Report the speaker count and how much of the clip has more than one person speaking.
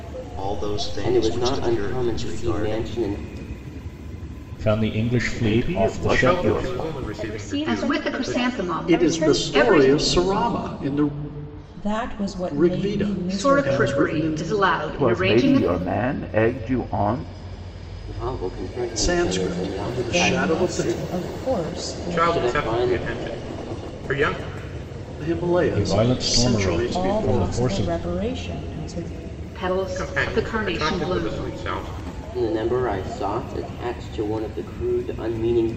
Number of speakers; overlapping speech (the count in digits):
9, about 48%